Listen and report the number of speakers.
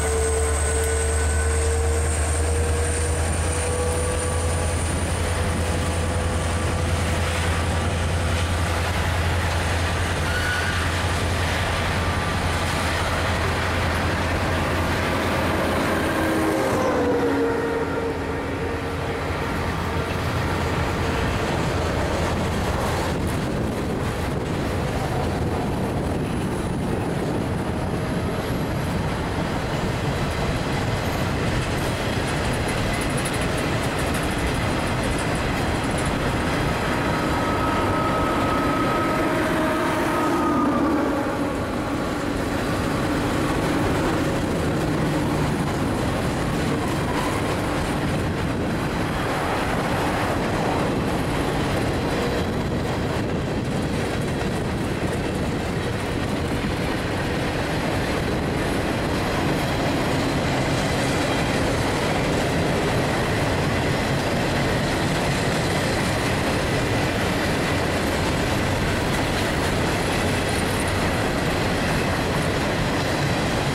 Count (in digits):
0